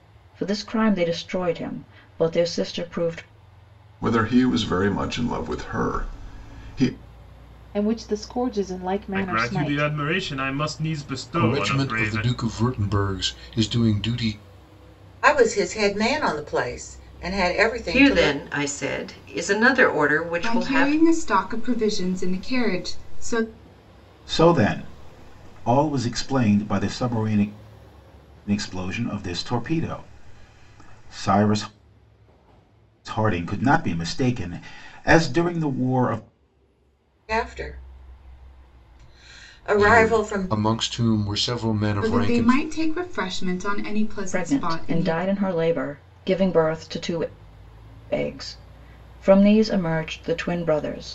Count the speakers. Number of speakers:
nine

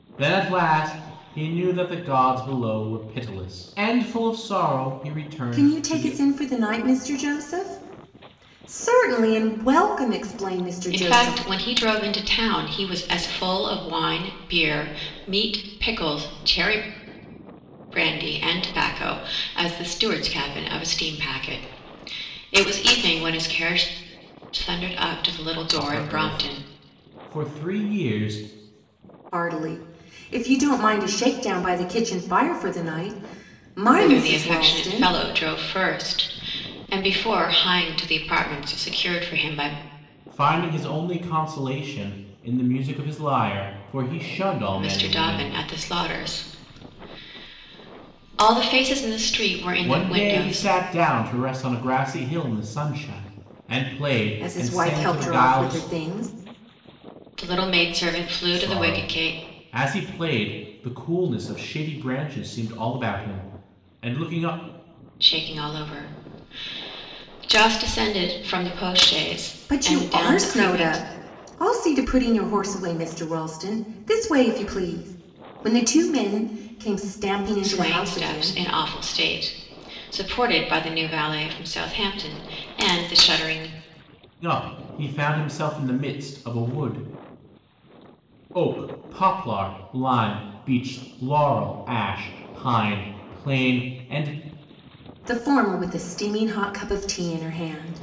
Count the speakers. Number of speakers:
three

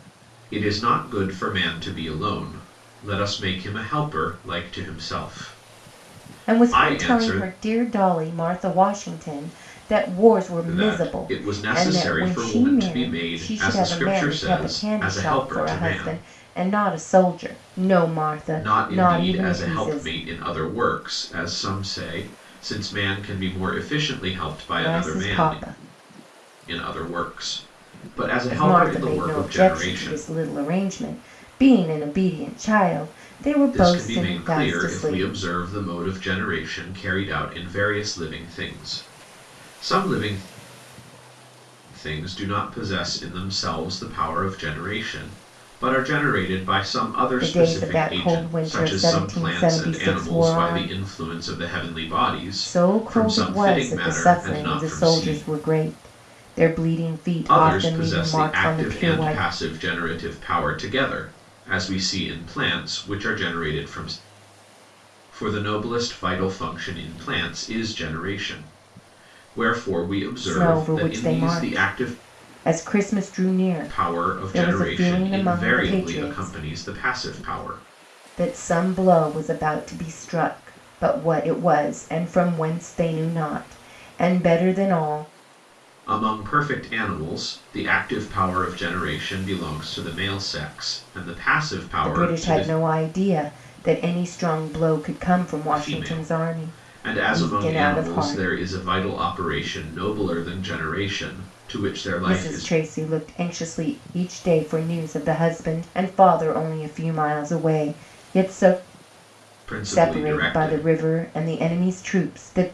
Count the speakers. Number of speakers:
two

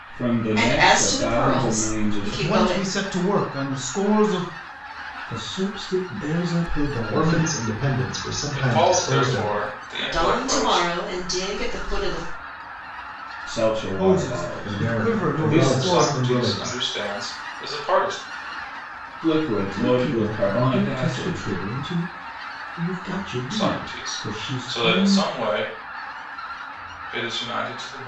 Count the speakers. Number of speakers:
six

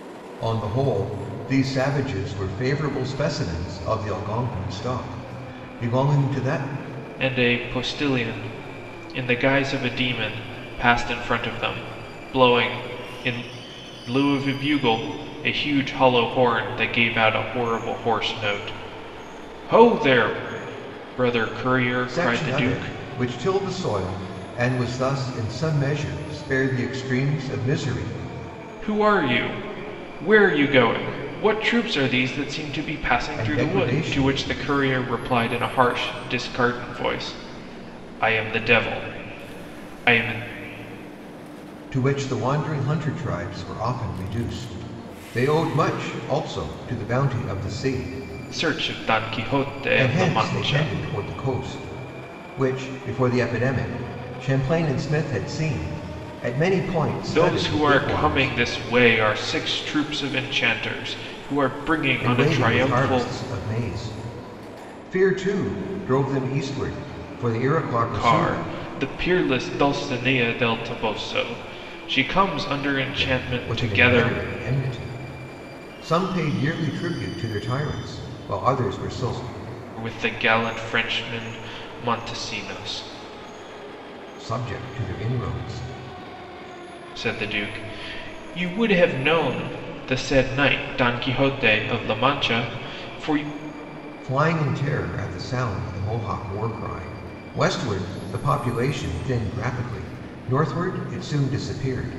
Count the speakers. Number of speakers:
two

